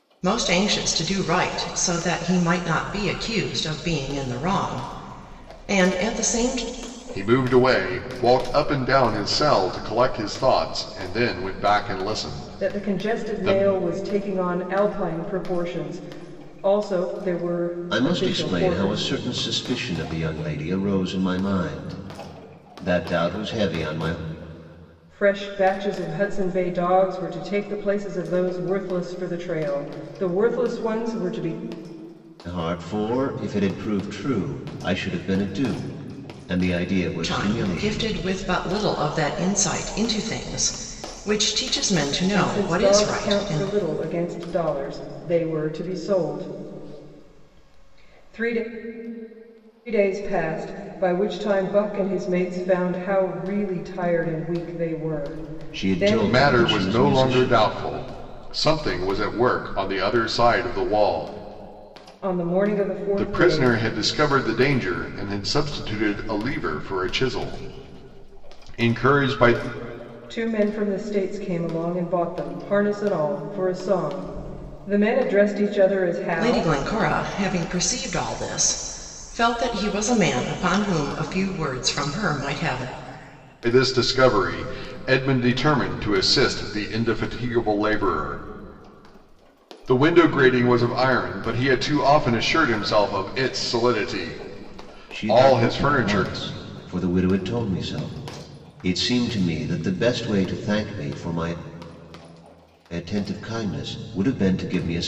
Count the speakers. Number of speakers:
4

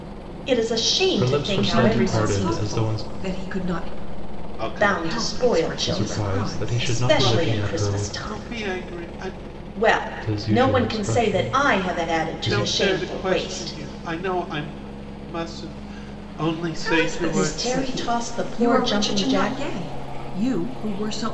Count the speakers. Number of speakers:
4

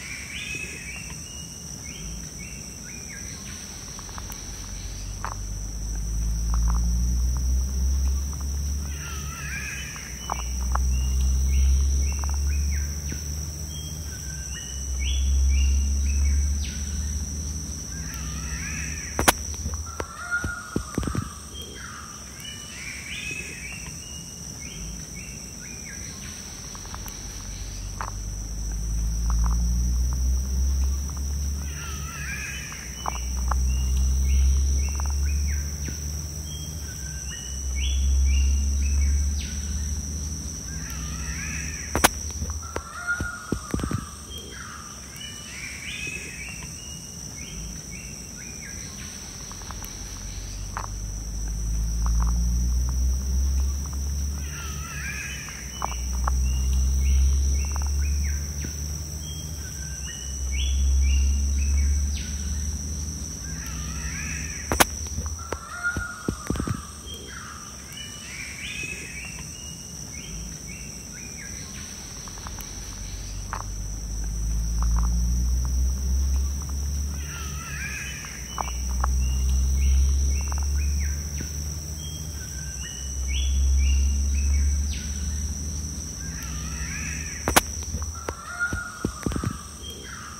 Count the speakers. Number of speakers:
0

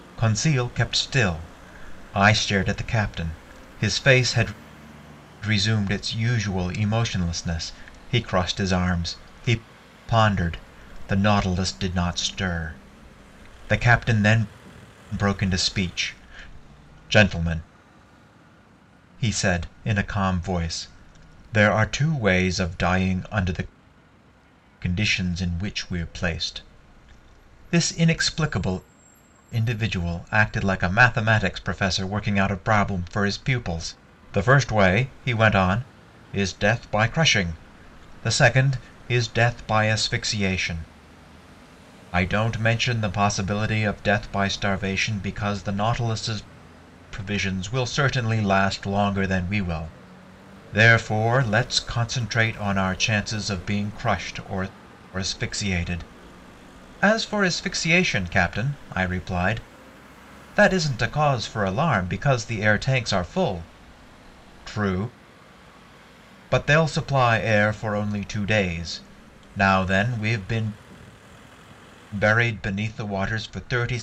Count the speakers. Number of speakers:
1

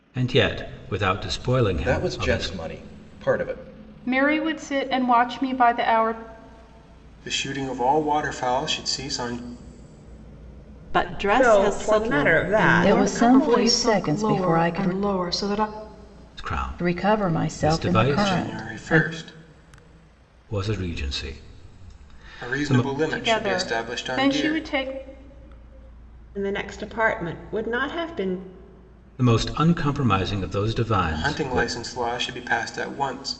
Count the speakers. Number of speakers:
8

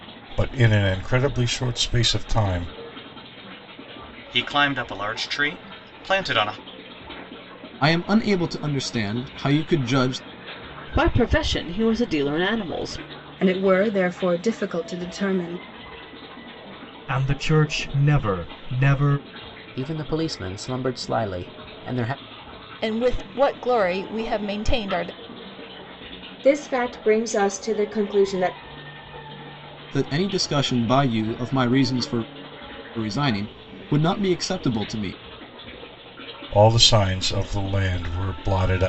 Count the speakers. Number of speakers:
9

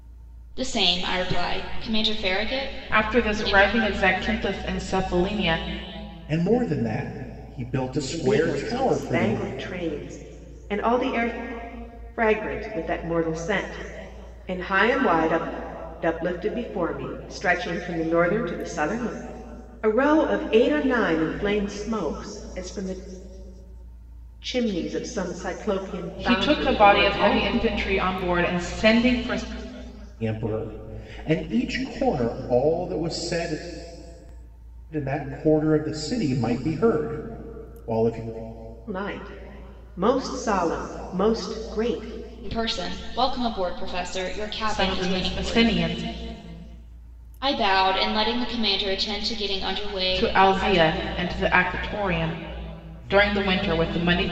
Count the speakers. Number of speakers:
4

